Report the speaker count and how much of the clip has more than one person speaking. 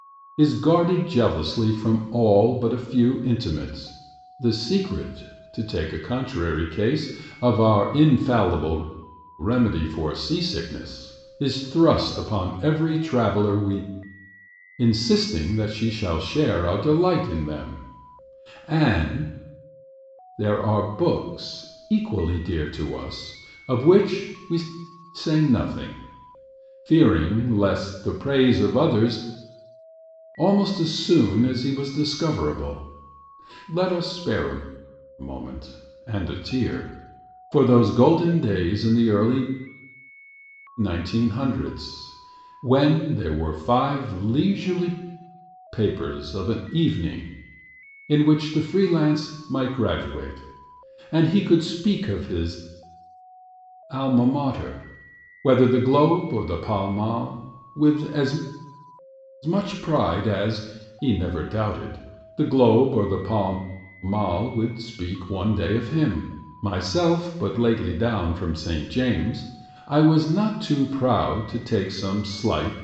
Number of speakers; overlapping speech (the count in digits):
1, no overlap